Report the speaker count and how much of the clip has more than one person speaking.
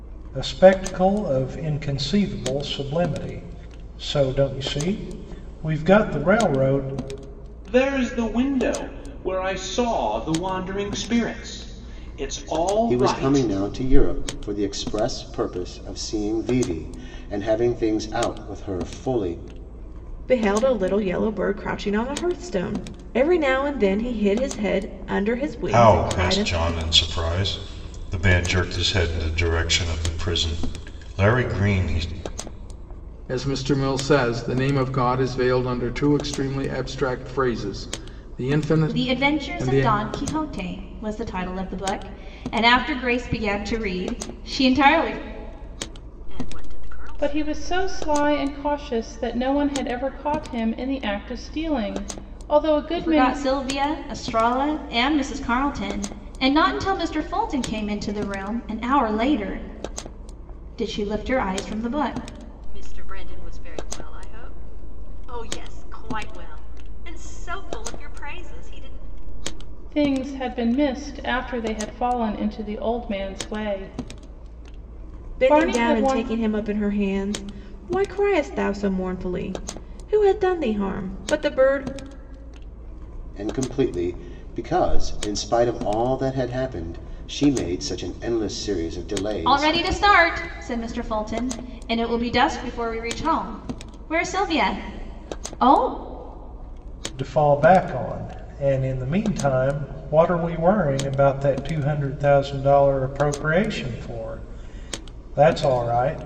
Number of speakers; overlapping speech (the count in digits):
9, about 4%